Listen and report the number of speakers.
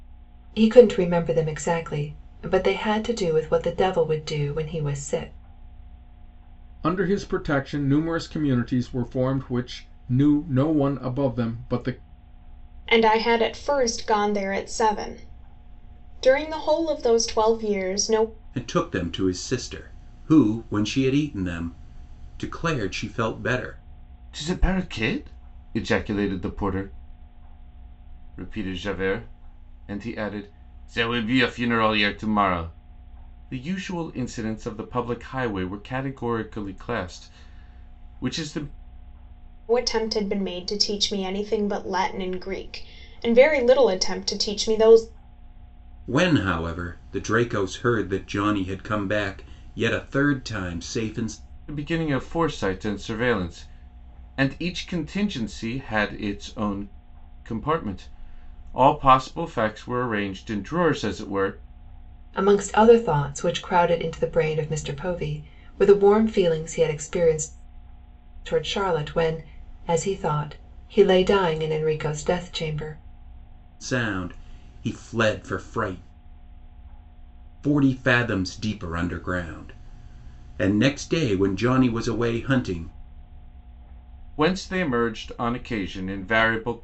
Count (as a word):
five